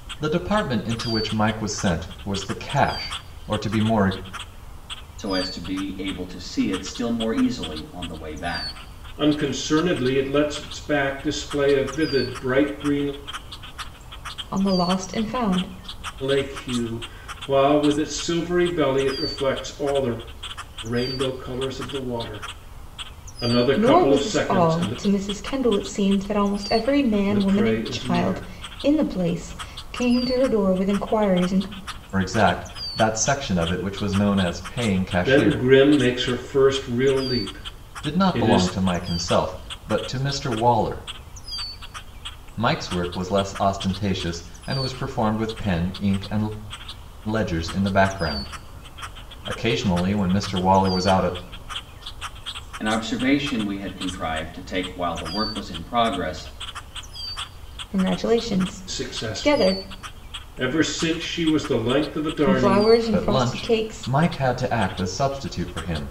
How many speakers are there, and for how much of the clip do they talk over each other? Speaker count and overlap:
four, about 9%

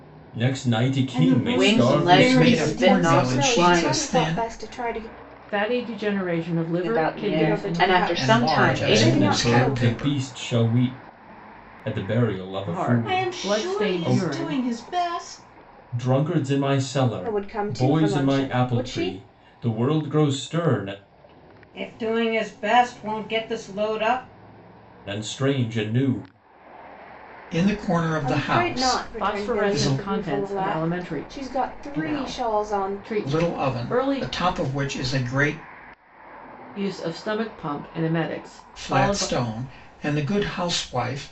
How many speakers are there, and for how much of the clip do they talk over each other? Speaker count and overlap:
six, about 39%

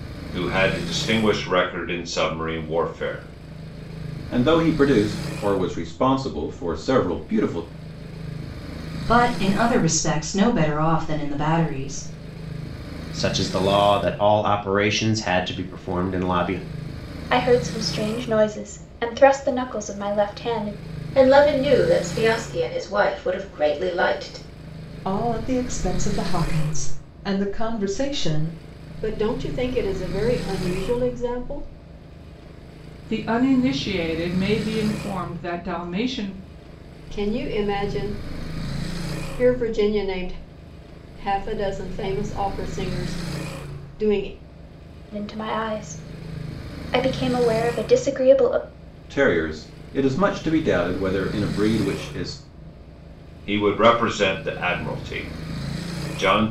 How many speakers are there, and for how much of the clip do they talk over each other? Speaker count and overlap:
nine, no overlap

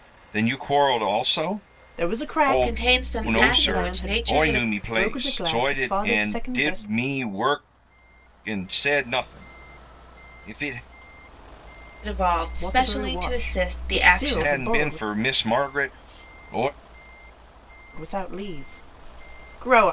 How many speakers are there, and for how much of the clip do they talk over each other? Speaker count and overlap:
three, about 37%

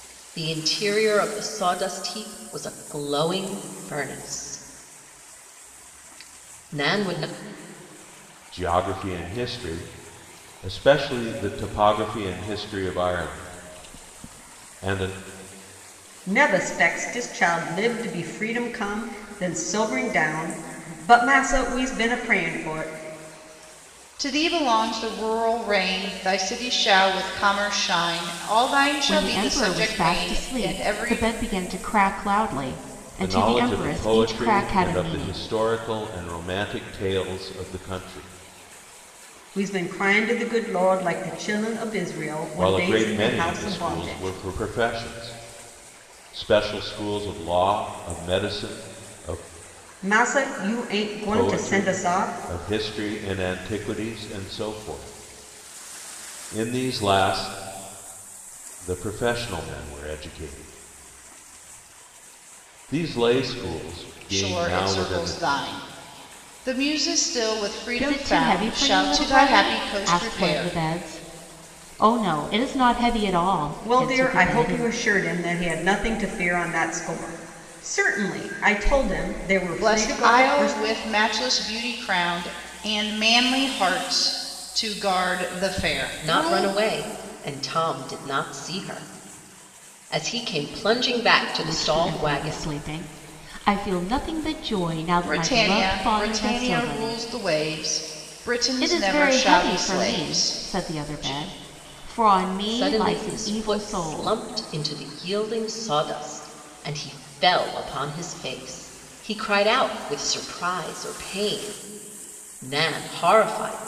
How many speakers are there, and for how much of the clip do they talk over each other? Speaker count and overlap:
five, about 19%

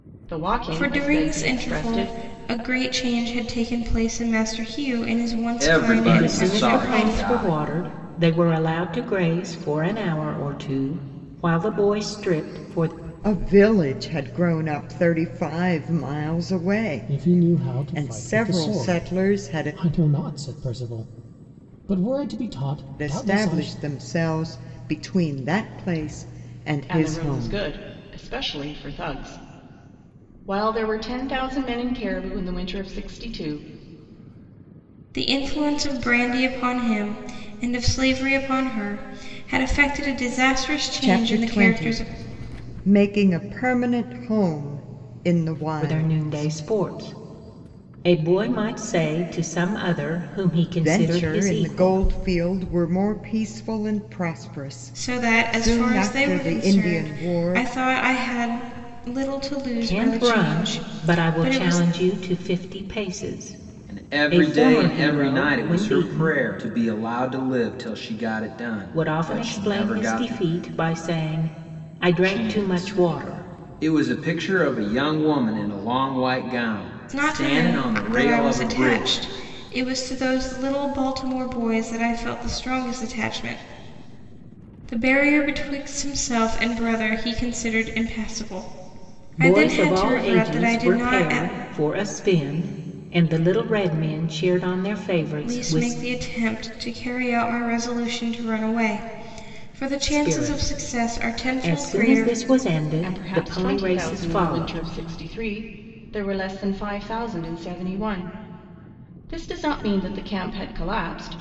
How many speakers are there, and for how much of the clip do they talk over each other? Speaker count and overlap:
six, about 27%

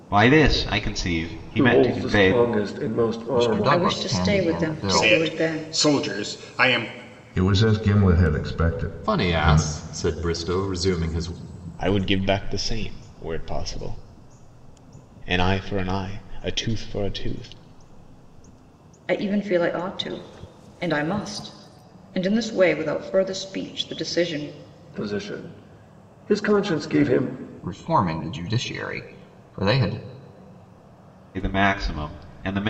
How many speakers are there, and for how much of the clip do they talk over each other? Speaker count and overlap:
eight, about 12%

